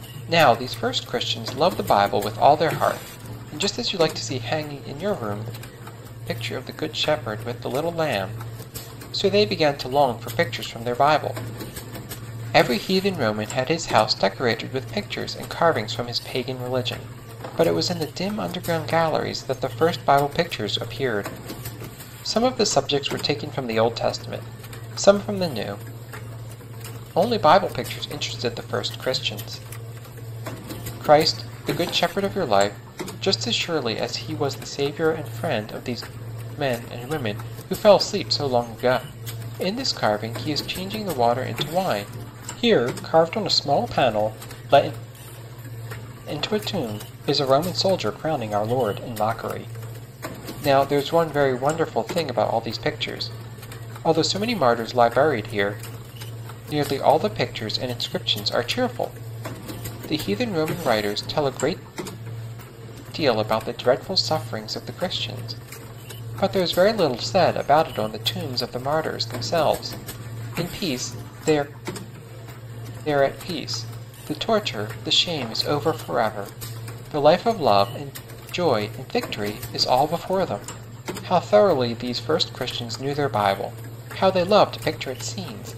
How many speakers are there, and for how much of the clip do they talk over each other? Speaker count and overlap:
1, no overlap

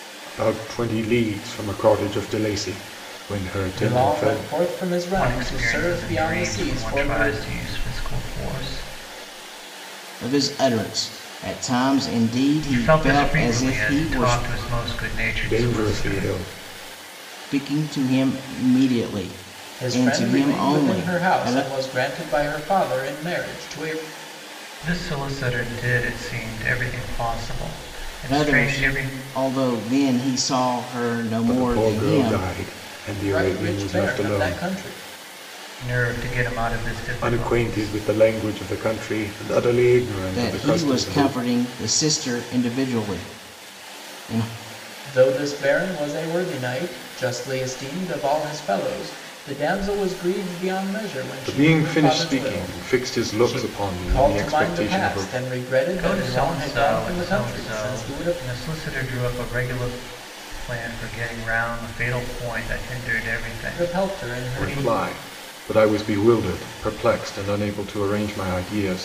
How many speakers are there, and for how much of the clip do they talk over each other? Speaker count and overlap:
4, about 29%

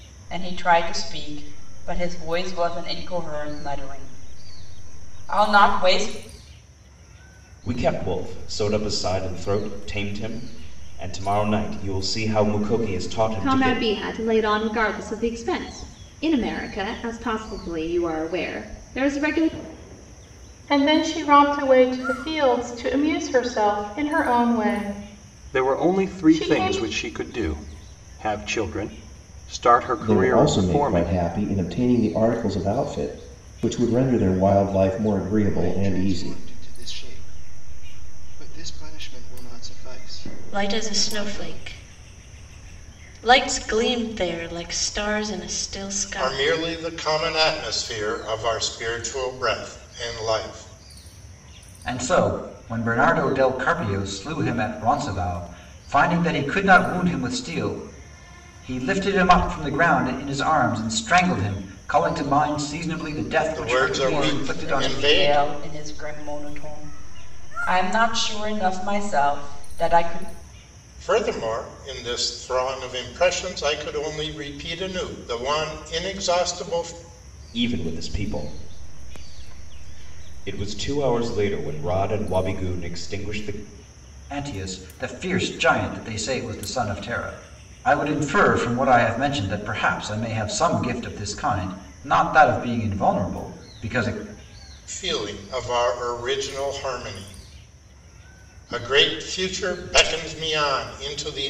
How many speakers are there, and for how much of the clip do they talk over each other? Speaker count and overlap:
10, about 8%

